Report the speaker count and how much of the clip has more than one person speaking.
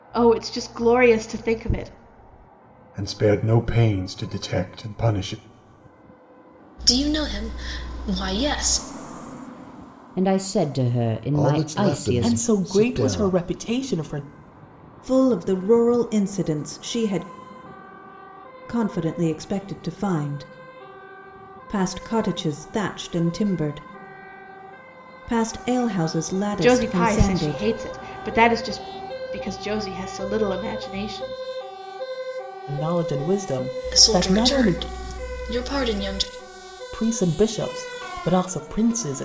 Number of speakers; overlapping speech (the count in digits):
7, about 11%